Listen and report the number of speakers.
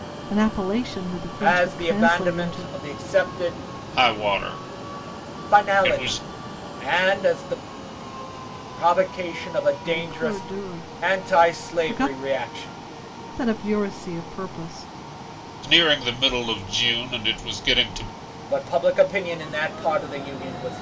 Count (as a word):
three